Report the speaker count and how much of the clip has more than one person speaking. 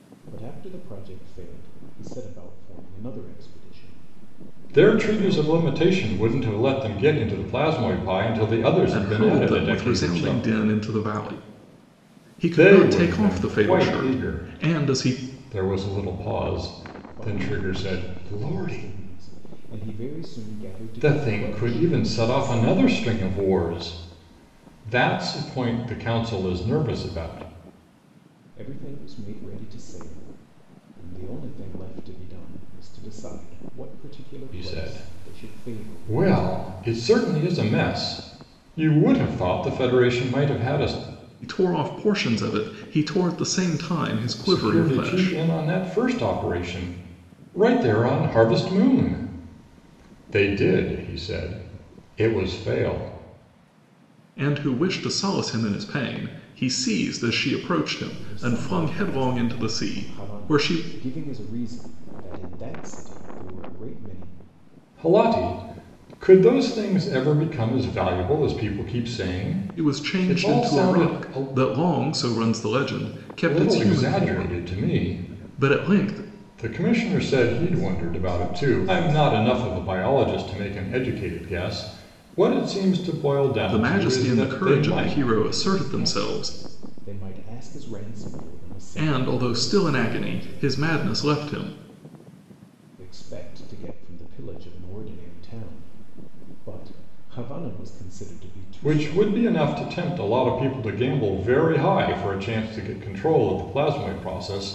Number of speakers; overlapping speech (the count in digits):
3, about 27%